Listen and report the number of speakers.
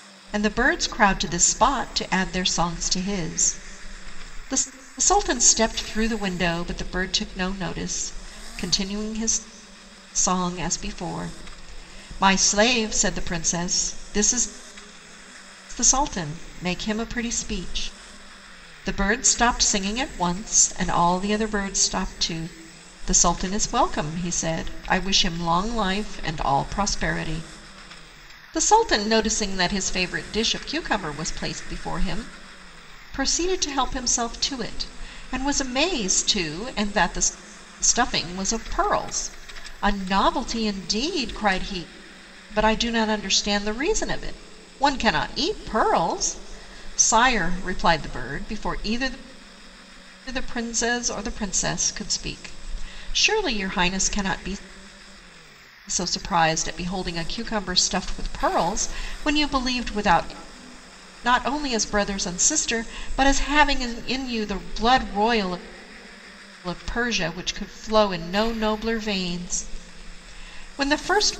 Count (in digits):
1